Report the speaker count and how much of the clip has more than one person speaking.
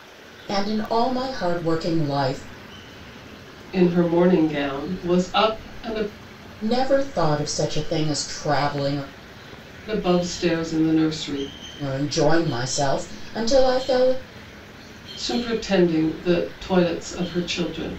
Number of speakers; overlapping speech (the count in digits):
2, no overlap